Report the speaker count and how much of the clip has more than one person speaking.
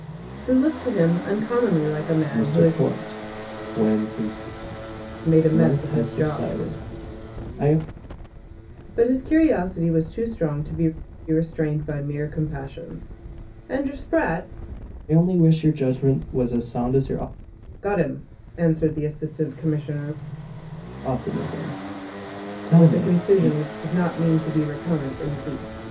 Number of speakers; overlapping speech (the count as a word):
two, about 10%